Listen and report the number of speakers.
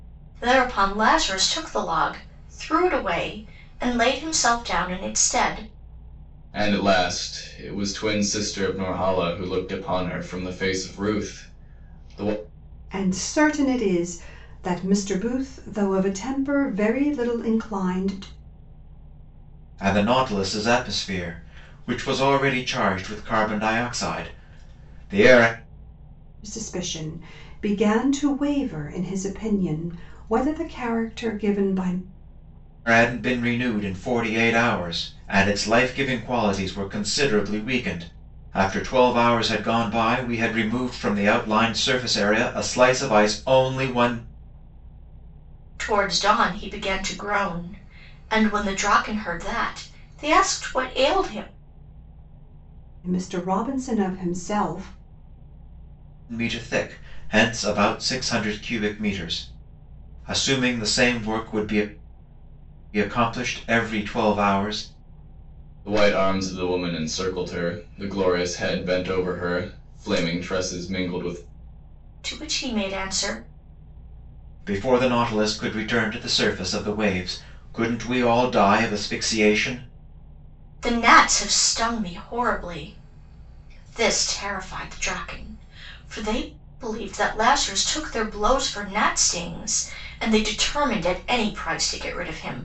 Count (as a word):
four